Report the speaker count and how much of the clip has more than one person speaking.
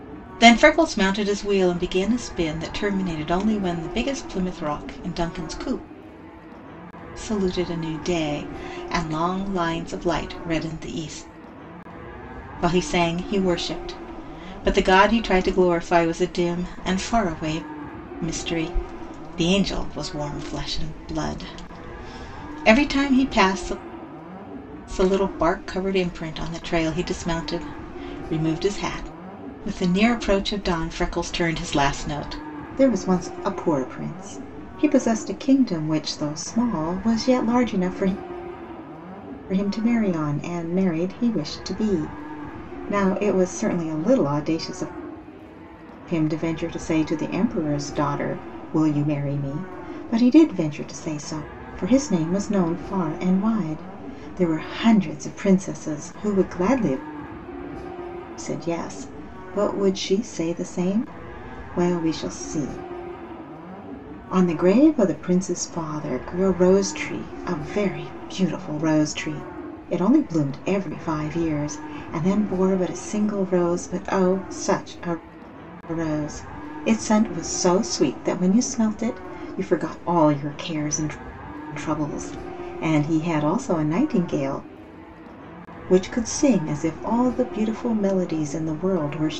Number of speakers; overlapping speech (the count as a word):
one, no overlap